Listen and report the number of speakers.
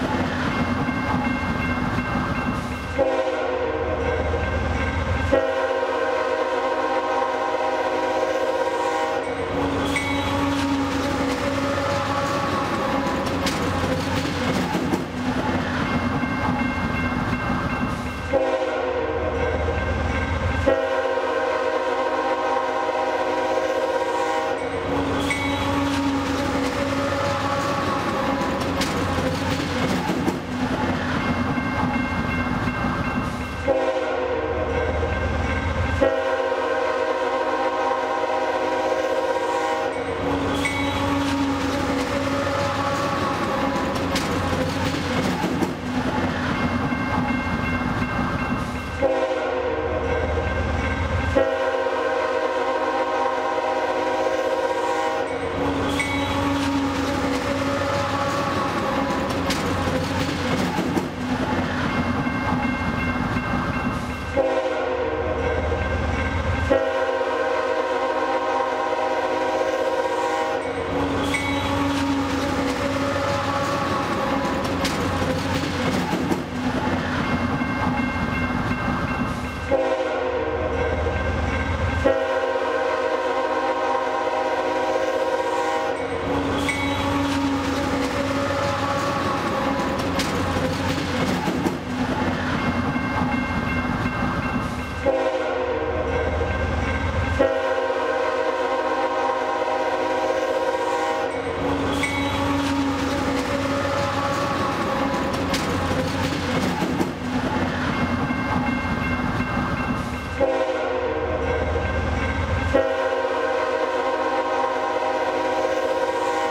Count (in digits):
0